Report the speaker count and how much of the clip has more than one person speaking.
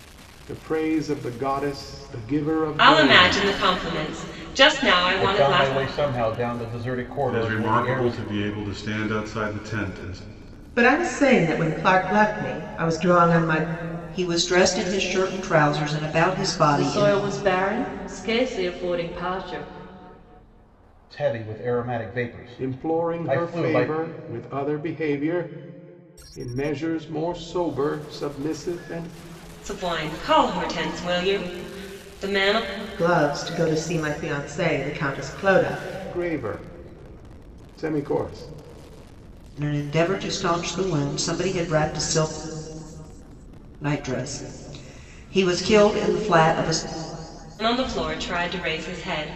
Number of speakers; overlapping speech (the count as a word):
seven, about 8%